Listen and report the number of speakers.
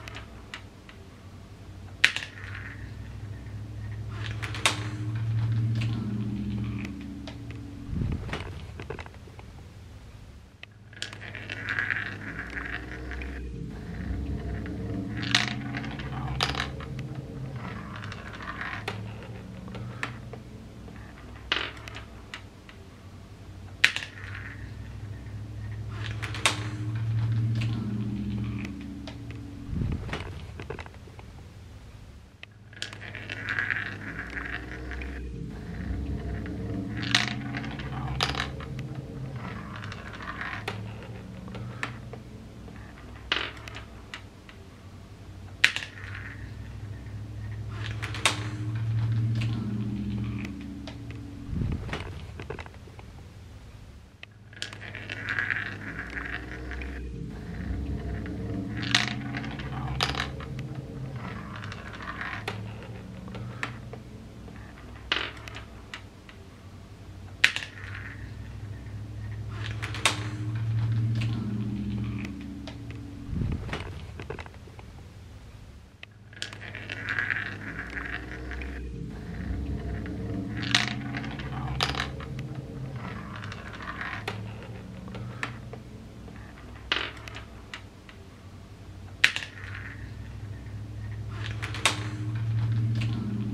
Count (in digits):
0